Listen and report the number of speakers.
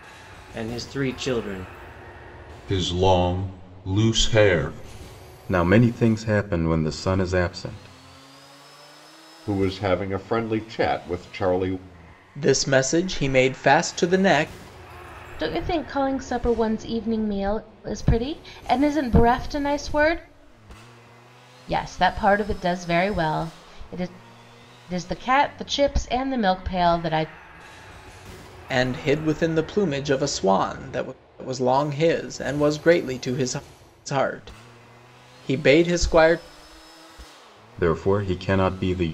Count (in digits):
6